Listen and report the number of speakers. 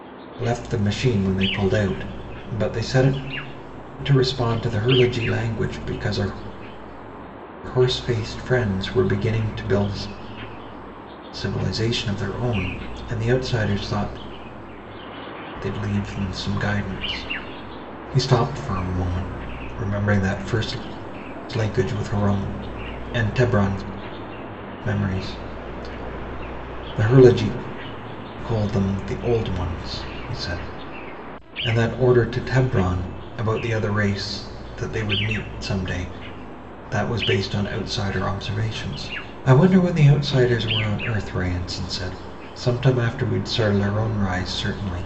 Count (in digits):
1